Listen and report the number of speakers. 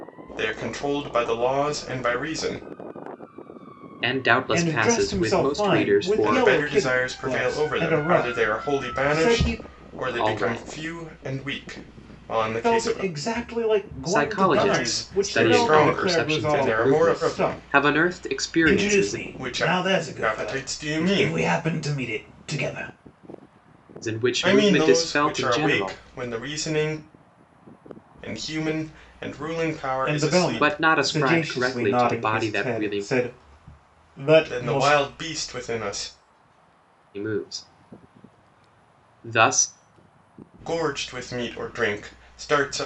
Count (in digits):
3